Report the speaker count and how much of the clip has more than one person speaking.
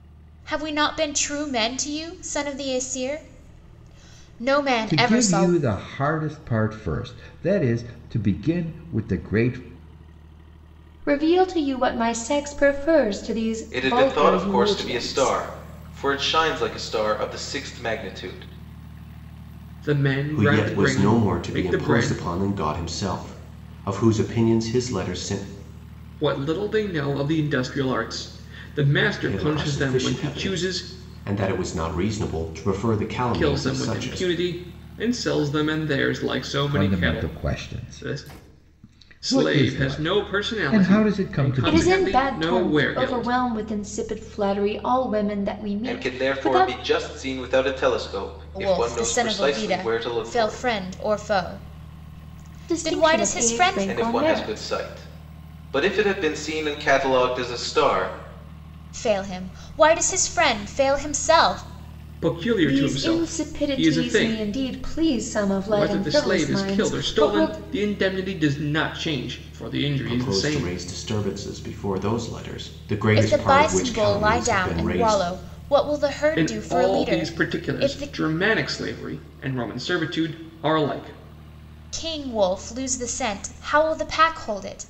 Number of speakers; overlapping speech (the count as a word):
six, about 31%